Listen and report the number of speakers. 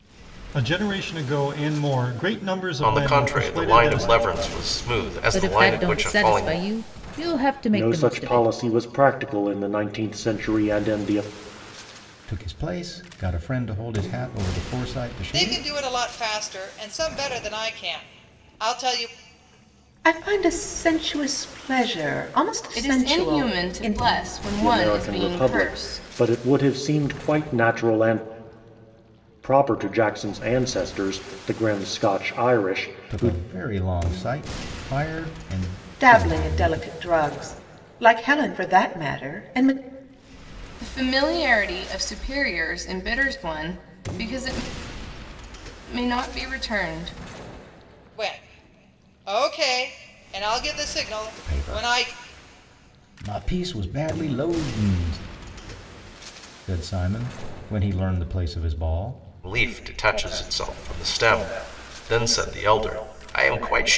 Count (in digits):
8